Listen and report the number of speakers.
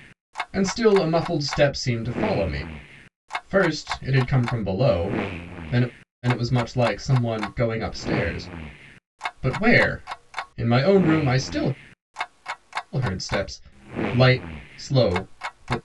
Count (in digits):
1